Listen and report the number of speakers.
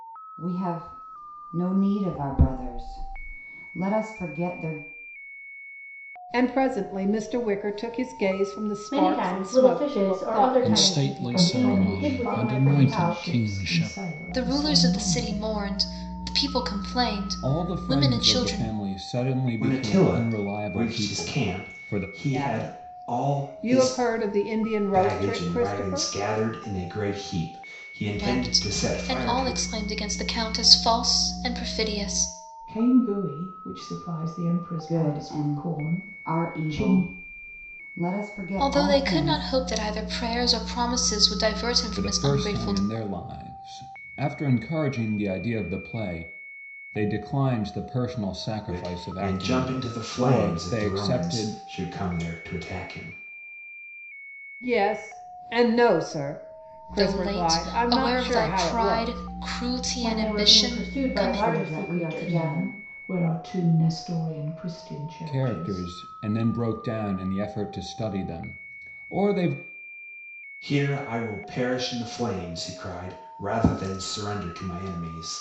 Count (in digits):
8